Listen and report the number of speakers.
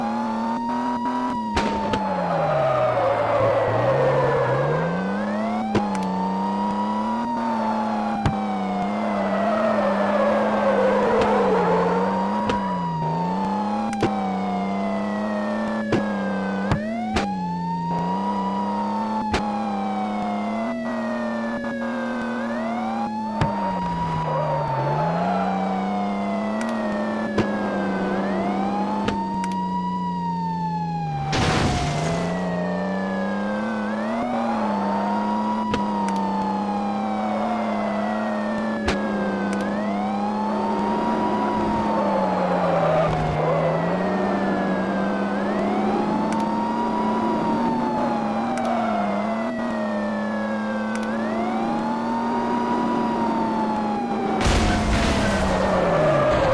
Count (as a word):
zero